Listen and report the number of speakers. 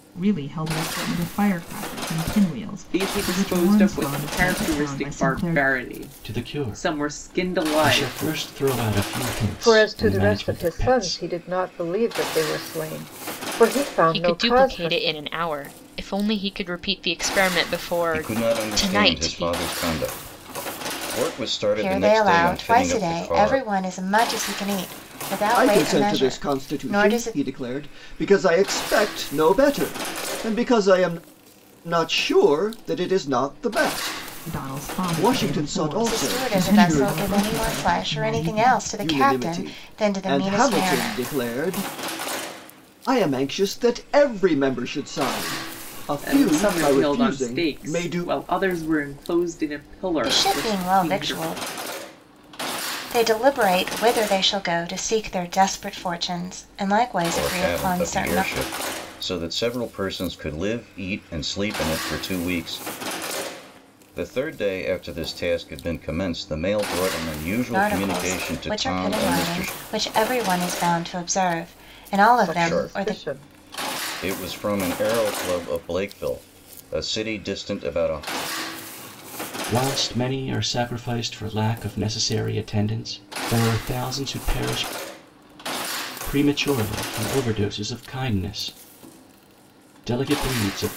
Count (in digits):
8